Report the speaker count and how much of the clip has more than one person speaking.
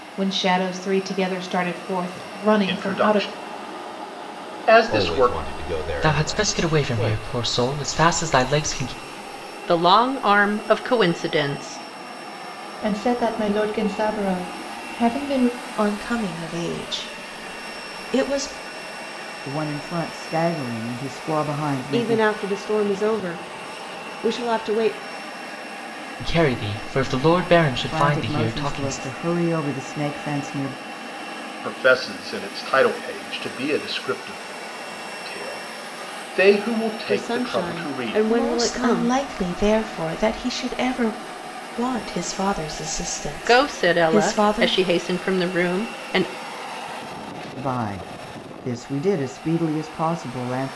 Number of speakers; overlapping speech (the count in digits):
9, about 15%